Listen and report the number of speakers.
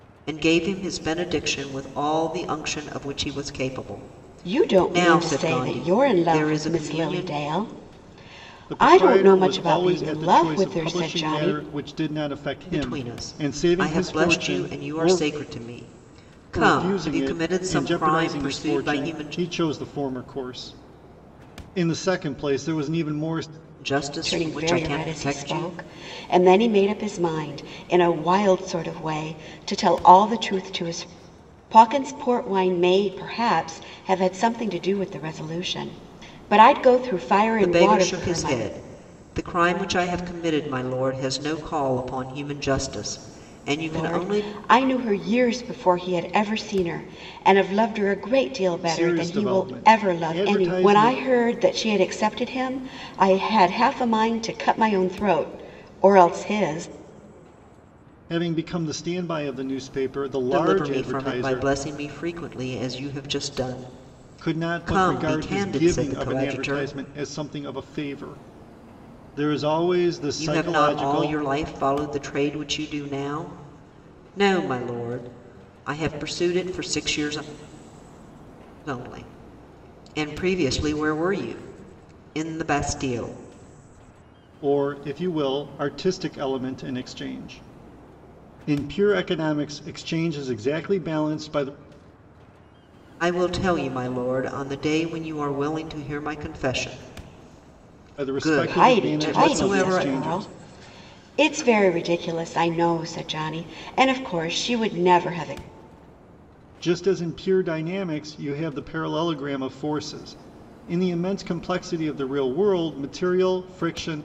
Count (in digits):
3